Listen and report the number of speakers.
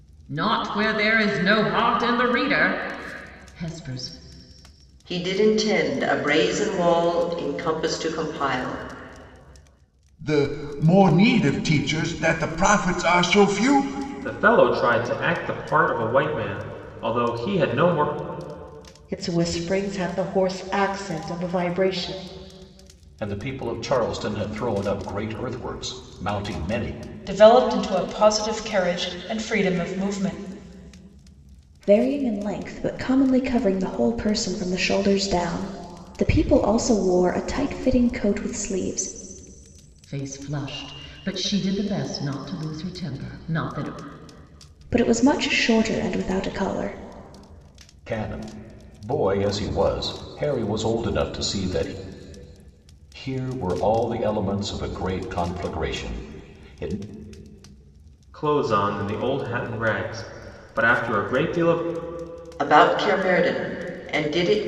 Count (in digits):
8